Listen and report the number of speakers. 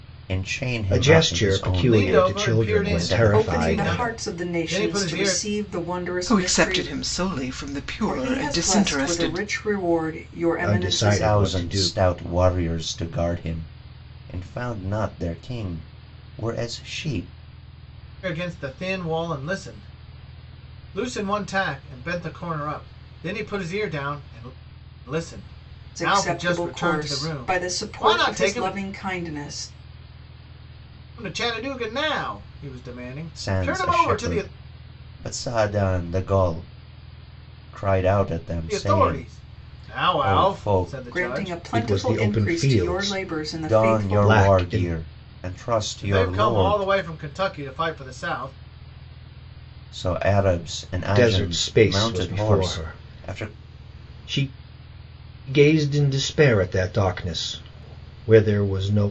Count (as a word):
five